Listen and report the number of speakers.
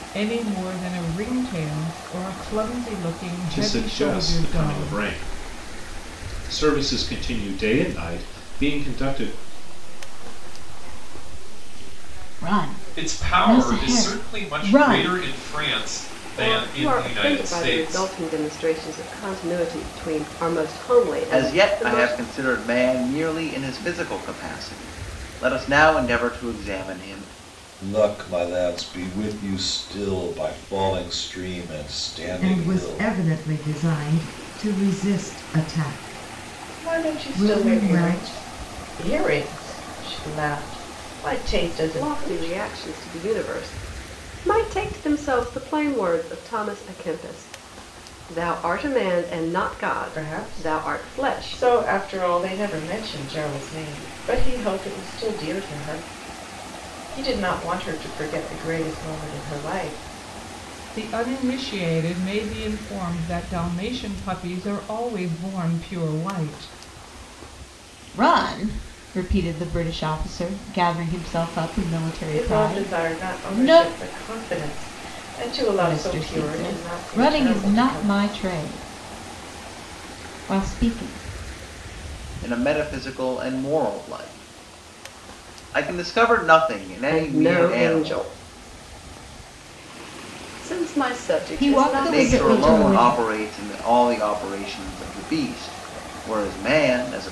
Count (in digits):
10